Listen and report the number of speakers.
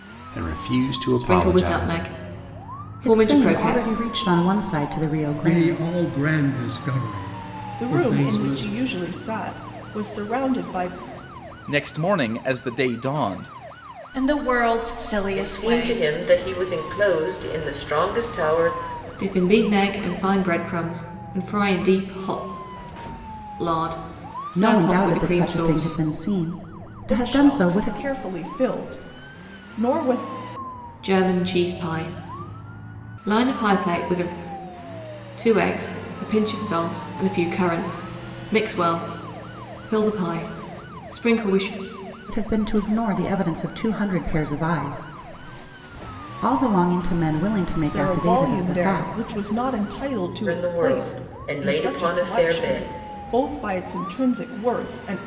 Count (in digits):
8